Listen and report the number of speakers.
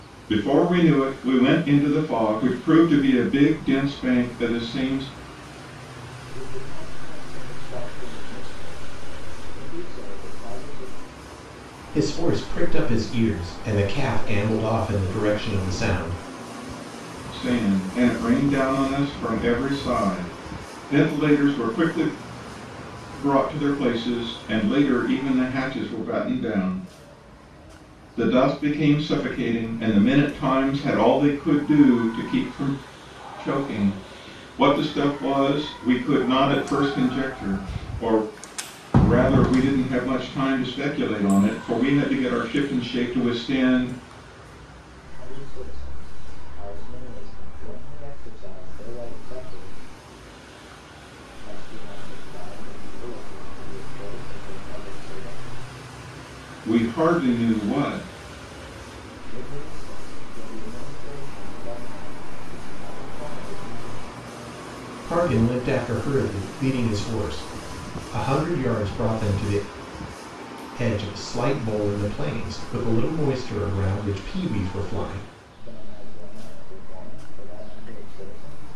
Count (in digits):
3